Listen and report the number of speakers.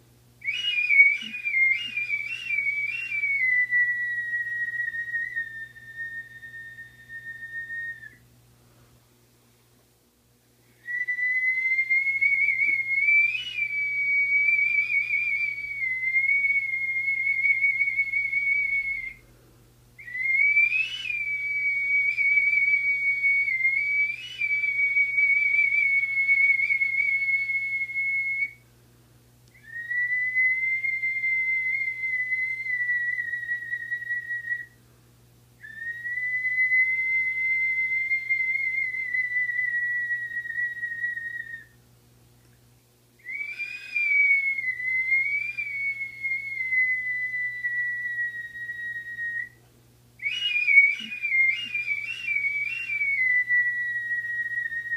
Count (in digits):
0